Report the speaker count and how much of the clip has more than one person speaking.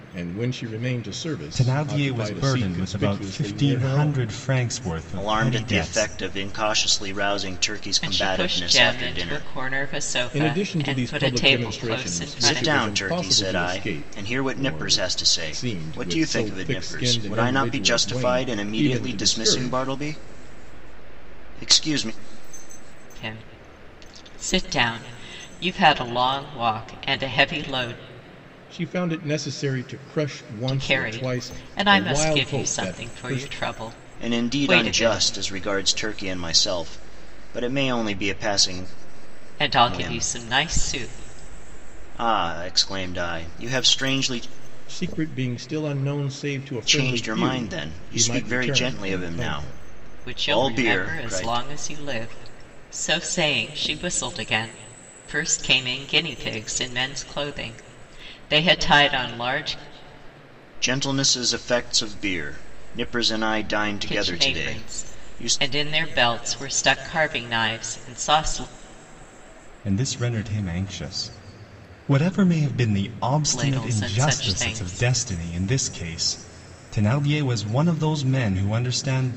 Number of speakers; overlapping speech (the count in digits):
4, about 35%